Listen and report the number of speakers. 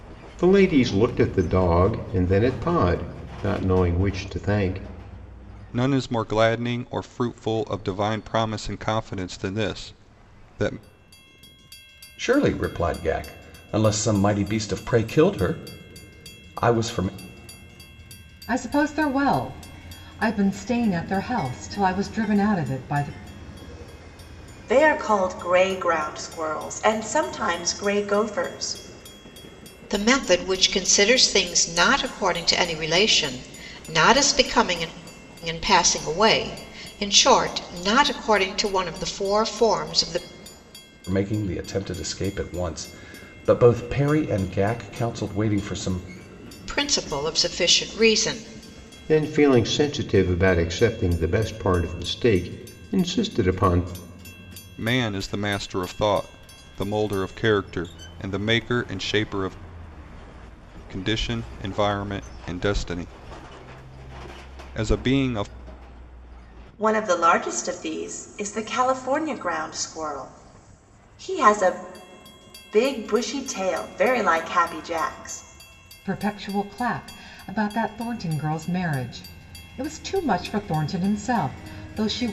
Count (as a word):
six